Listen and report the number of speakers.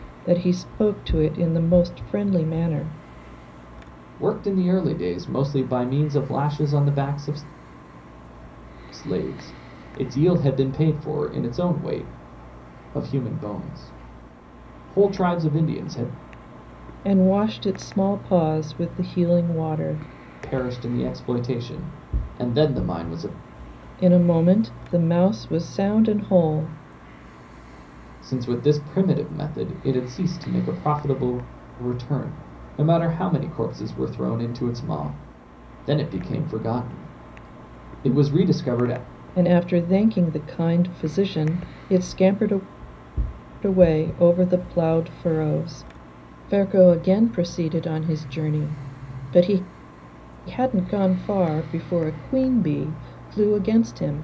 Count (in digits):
2